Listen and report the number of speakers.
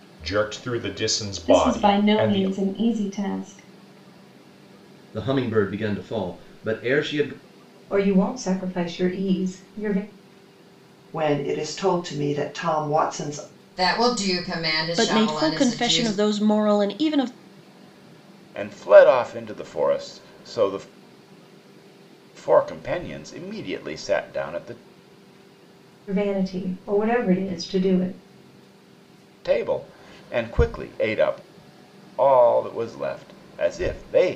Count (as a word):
eight